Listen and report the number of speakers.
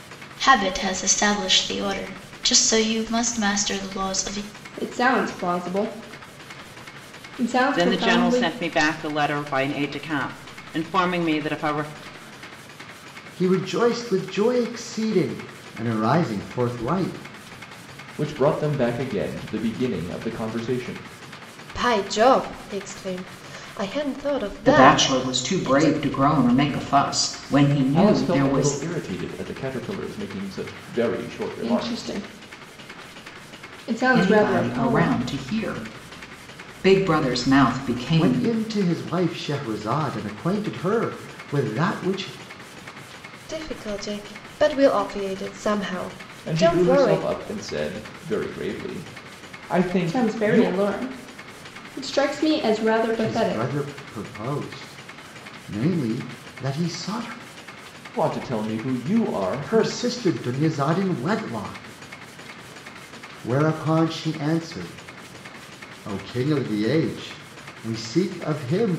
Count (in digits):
7